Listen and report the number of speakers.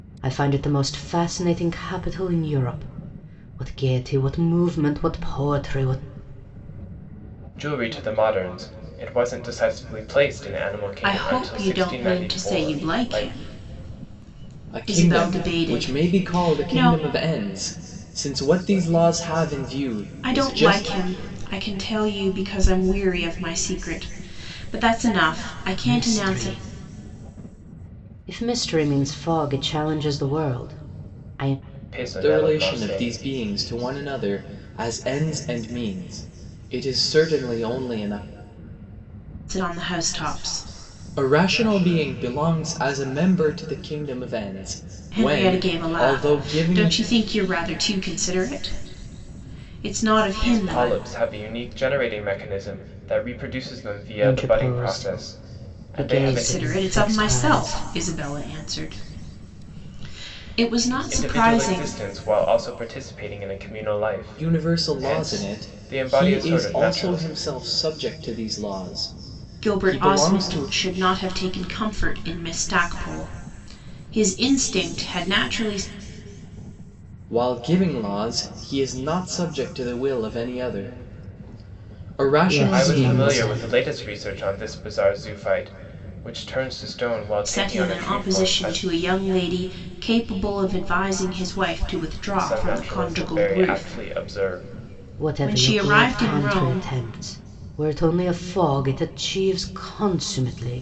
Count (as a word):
four